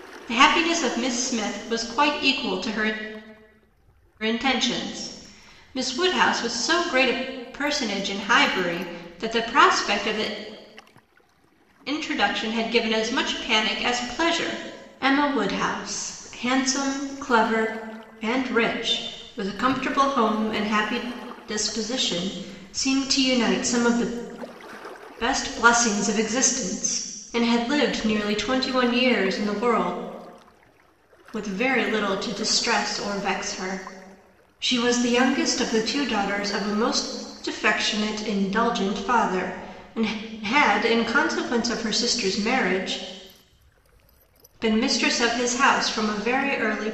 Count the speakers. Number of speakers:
1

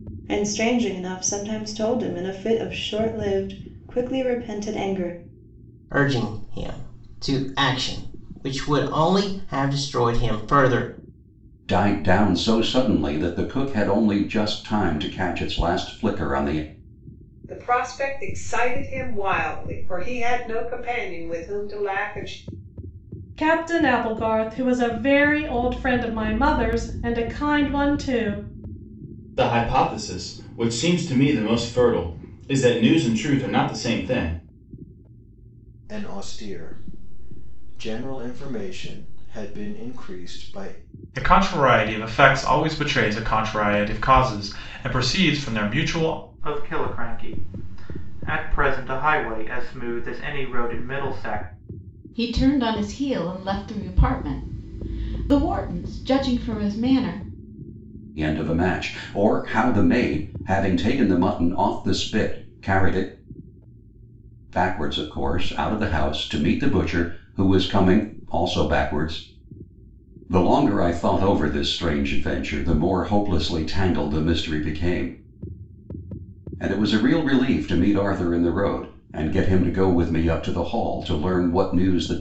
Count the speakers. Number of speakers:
10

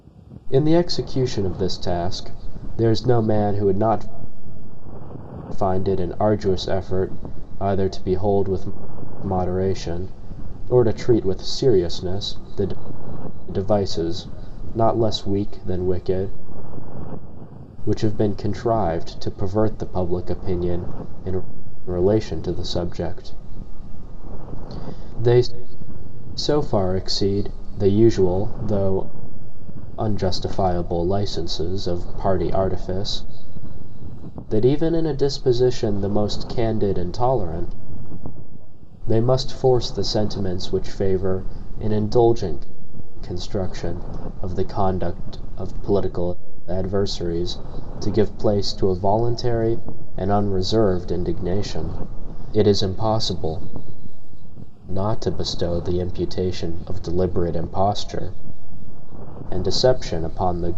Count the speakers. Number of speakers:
1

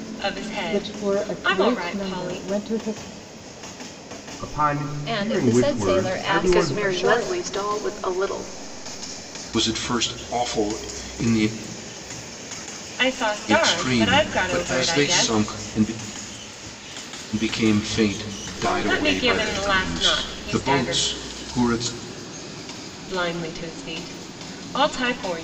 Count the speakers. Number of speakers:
6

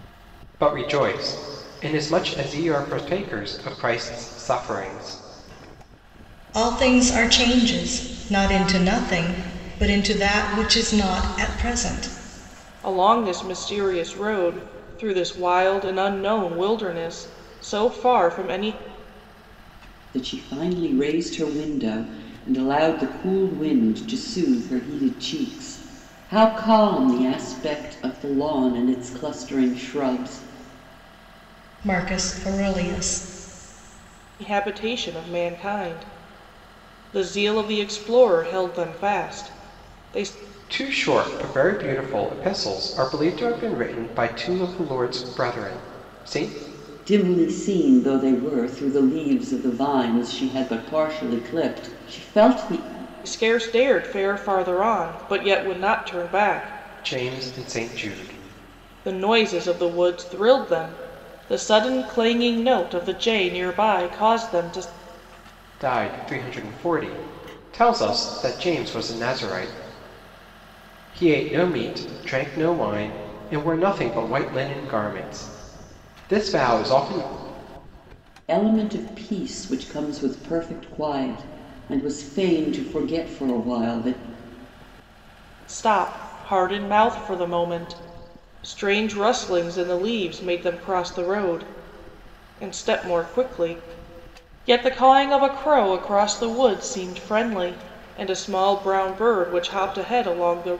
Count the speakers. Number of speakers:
4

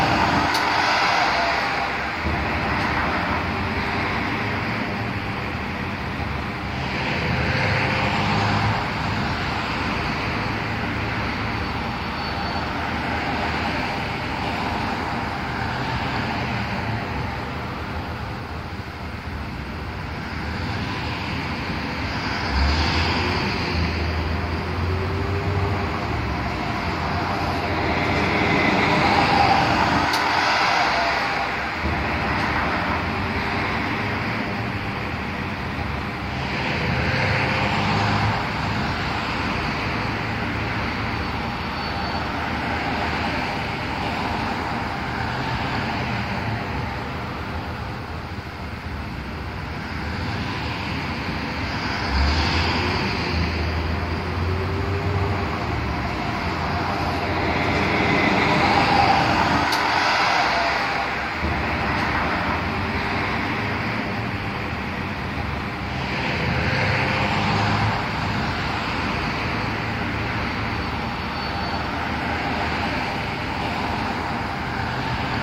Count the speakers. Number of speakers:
0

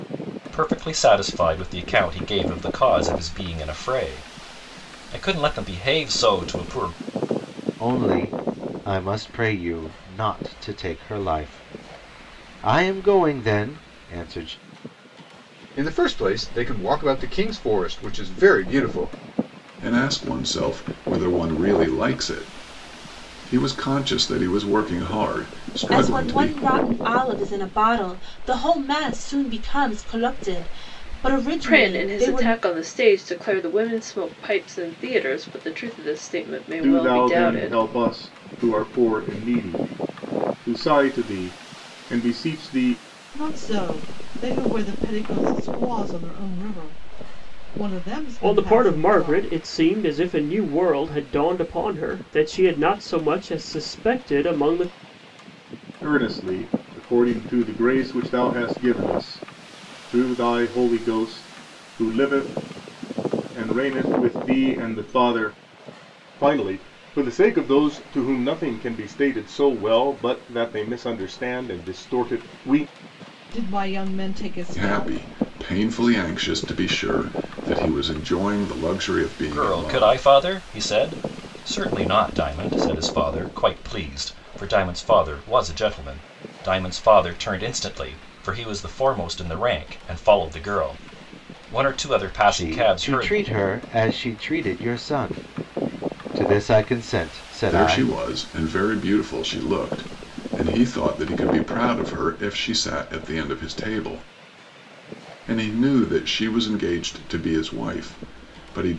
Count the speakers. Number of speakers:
9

